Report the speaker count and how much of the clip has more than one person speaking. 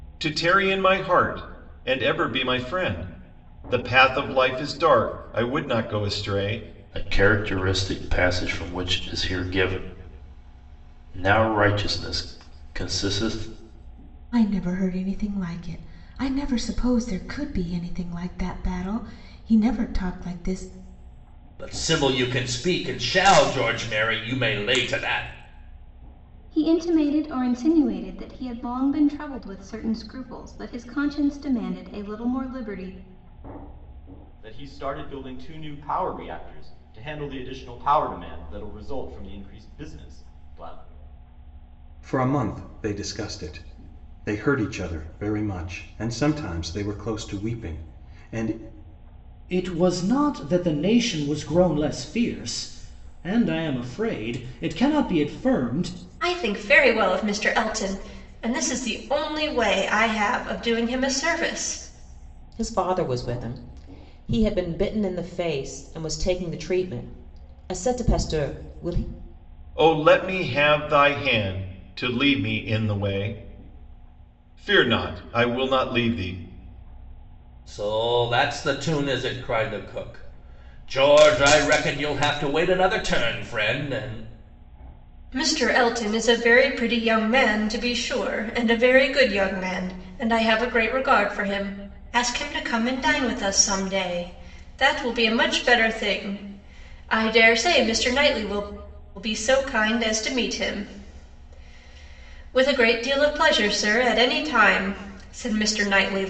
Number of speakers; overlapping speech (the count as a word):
ten, no overlap